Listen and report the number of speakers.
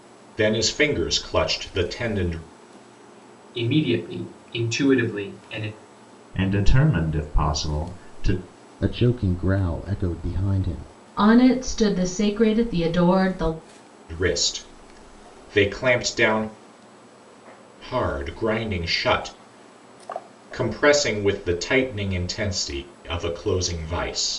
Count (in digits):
5